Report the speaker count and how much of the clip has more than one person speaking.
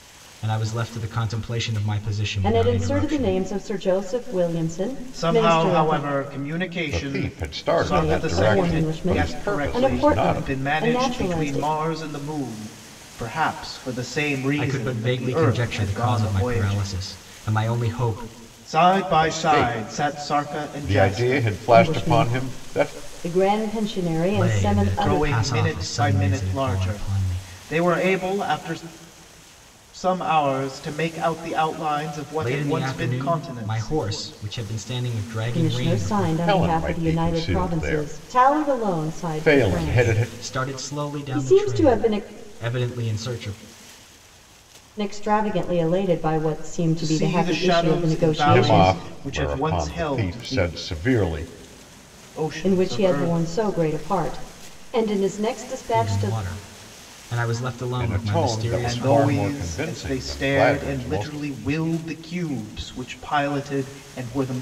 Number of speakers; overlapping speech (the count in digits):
4, about 51%